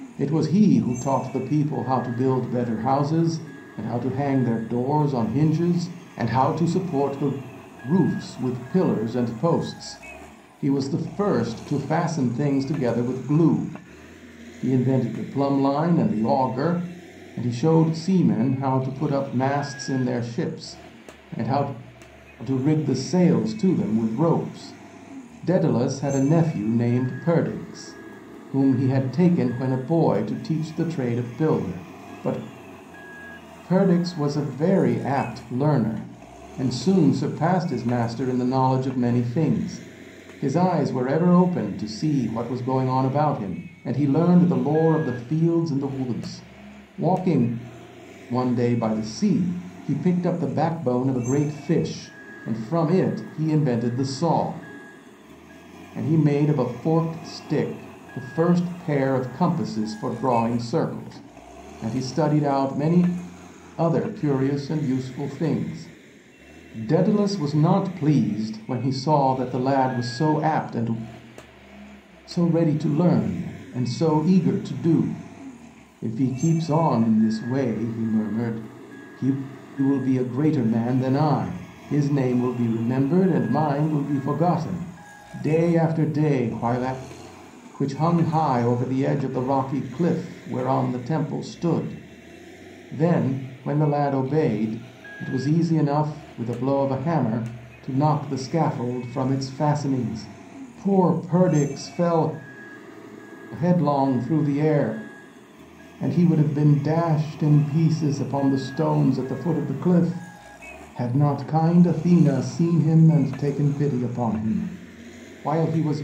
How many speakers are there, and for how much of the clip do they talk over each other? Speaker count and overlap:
1, no overlap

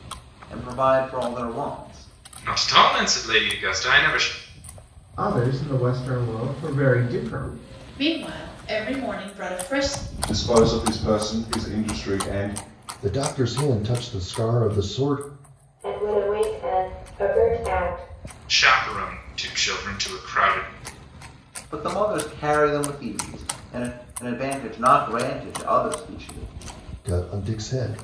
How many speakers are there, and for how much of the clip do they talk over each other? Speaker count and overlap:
7, no overlap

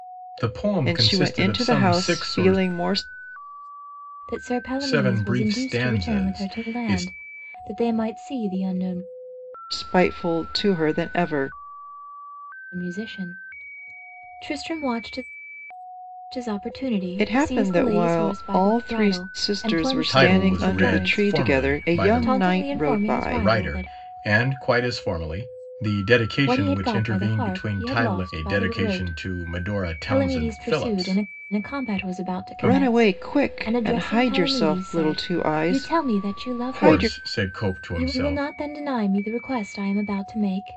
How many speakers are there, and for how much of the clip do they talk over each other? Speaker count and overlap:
3, about 54%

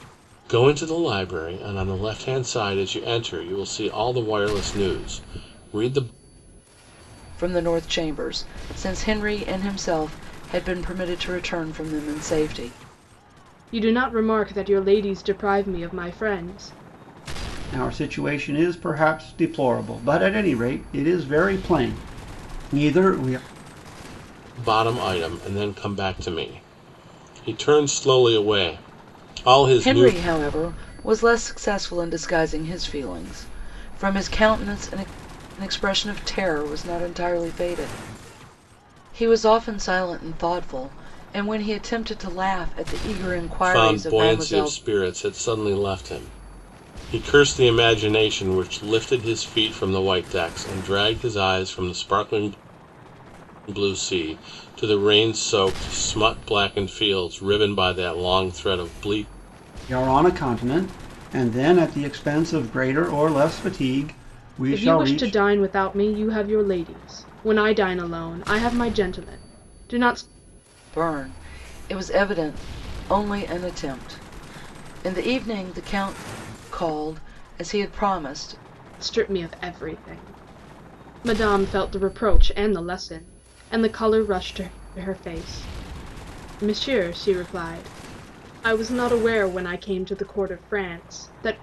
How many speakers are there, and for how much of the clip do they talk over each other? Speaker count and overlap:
4, about 2%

